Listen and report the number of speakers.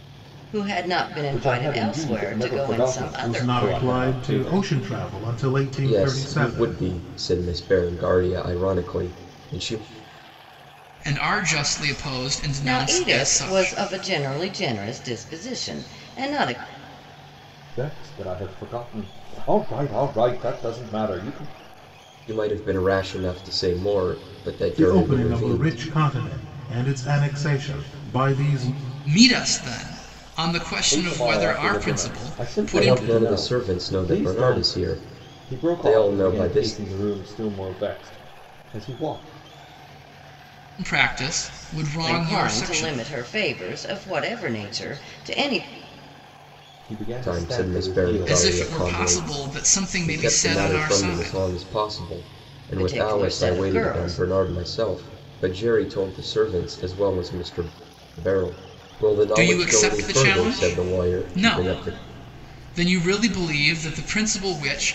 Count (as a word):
five